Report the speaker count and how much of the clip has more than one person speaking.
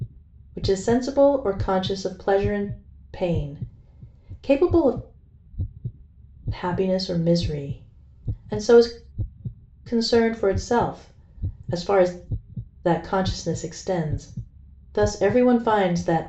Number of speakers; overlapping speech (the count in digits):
1, no overlap